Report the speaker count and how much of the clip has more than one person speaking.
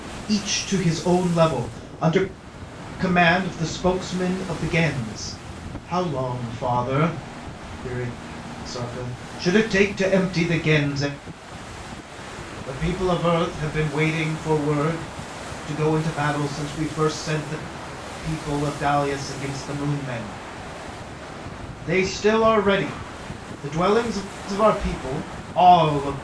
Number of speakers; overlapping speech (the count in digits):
1, no overlap